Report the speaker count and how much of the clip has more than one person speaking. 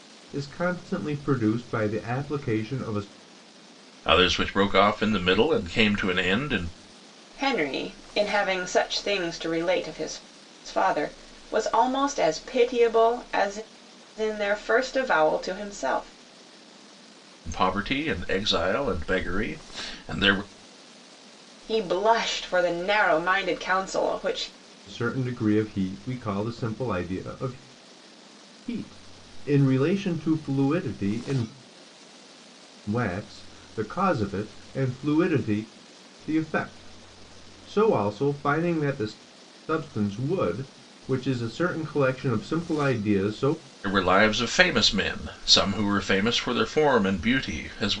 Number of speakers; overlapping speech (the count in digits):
3, no overlap